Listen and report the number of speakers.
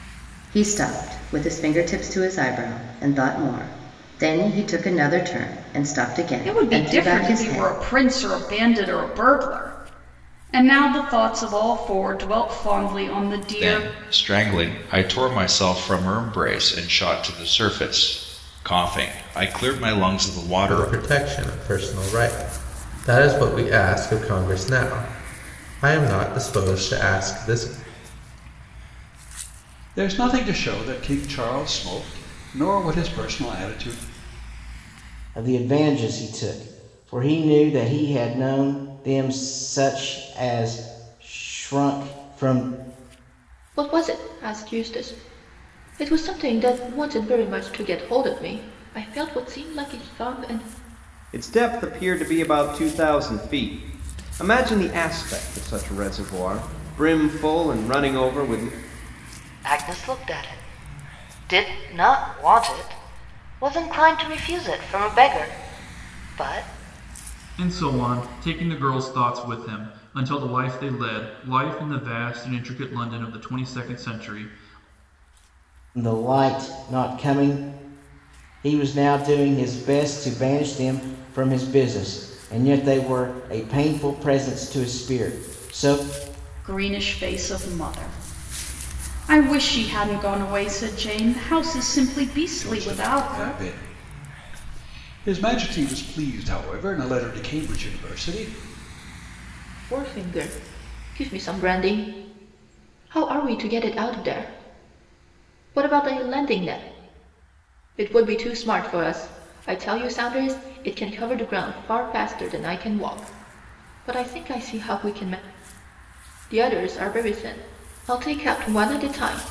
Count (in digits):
10